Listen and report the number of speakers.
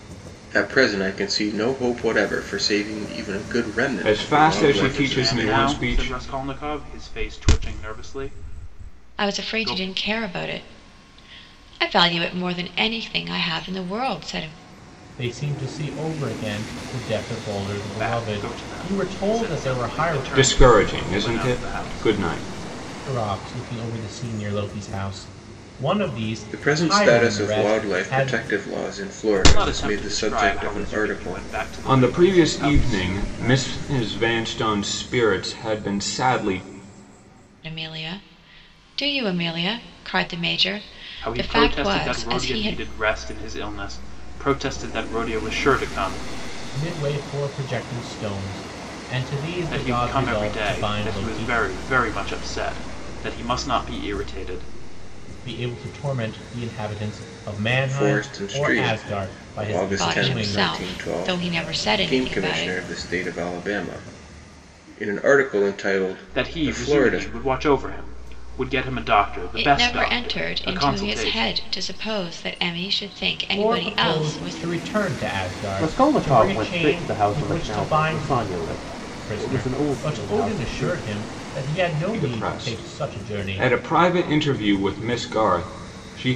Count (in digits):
5